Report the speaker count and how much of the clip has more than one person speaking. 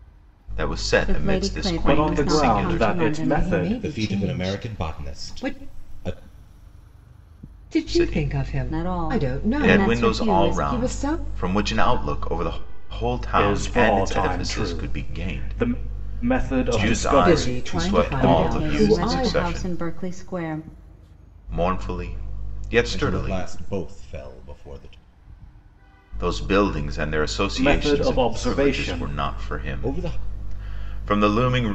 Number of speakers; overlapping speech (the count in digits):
5, about 54%